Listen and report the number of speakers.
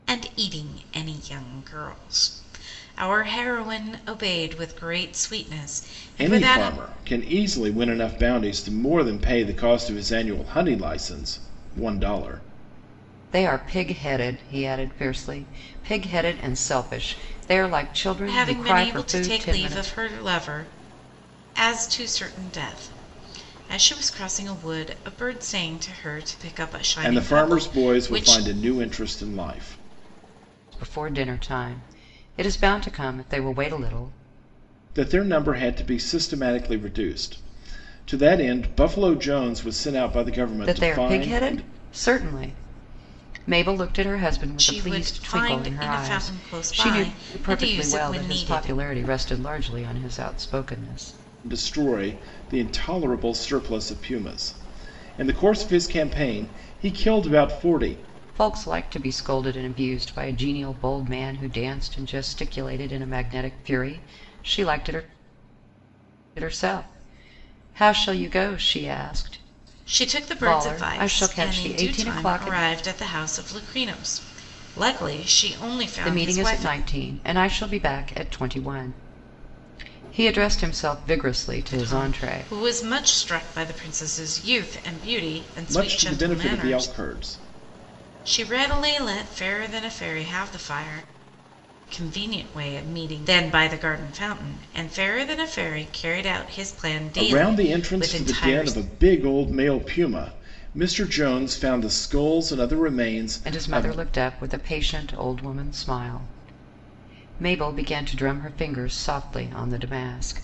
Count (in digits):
3